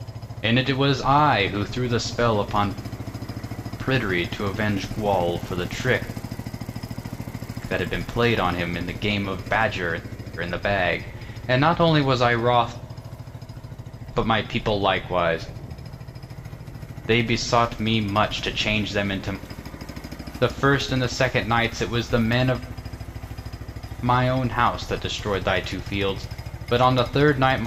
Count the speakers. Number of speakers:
1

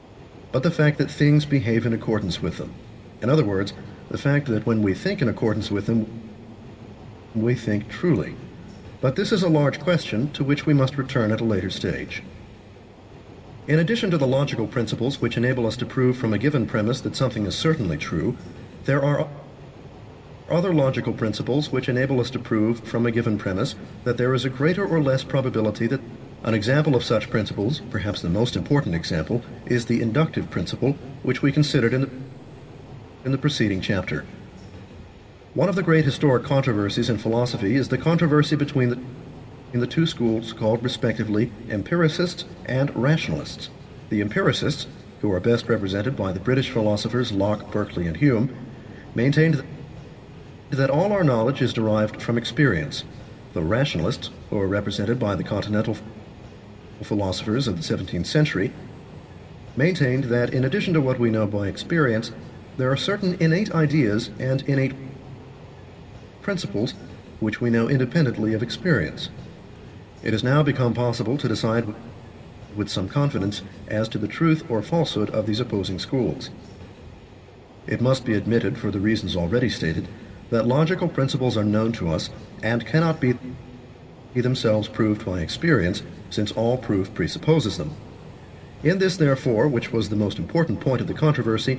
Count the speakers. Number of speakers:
1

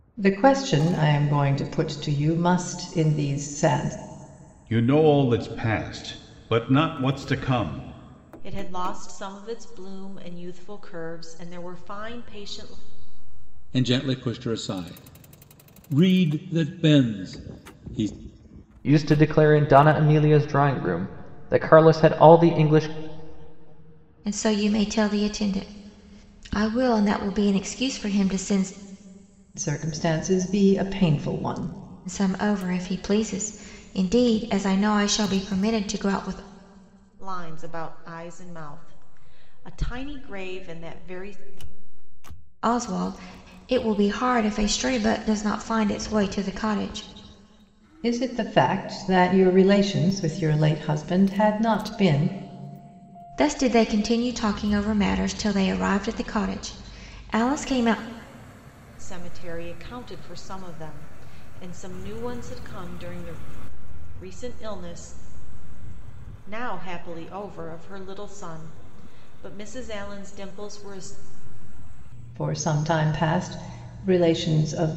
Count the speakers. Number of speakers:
6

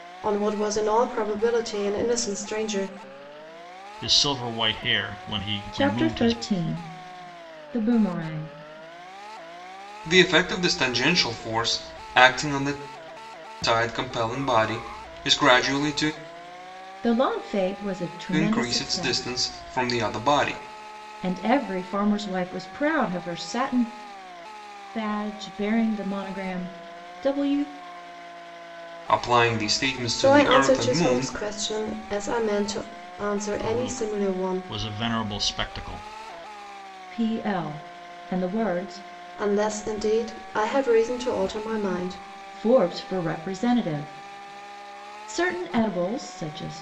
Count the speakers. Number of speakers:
4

